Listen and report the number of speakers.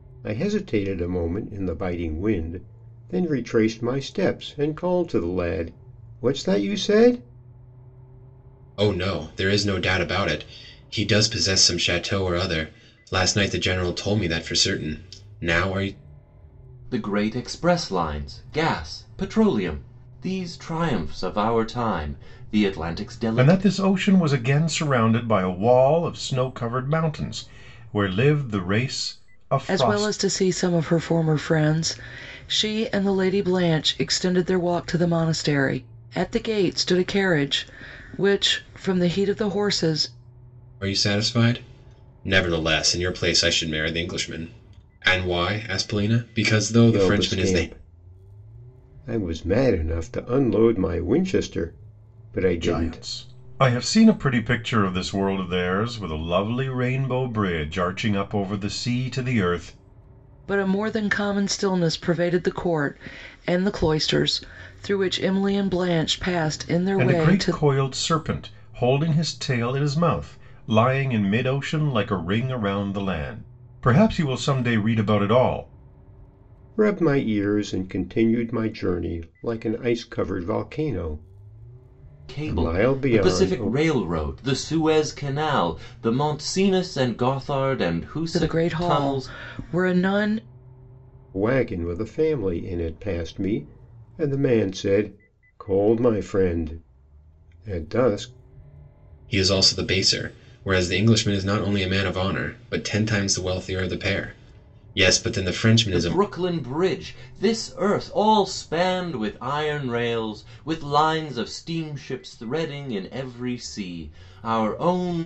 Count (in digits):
5